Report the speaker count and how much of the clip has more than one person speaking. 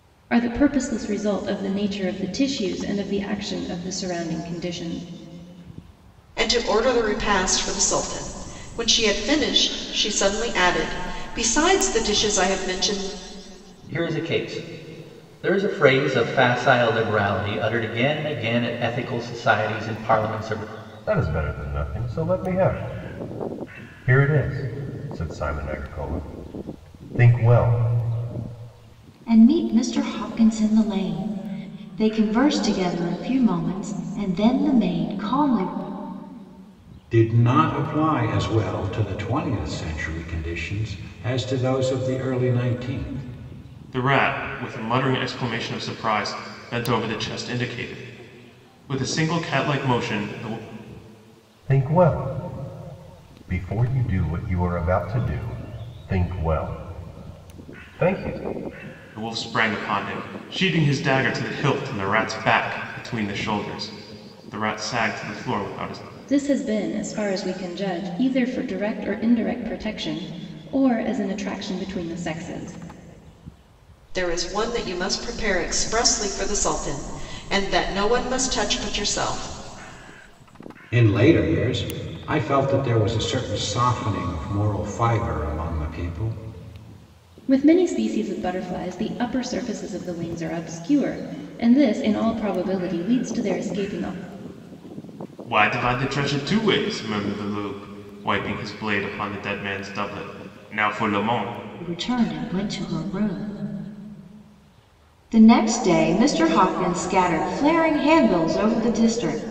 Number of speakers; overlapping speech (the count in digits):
7, no overlap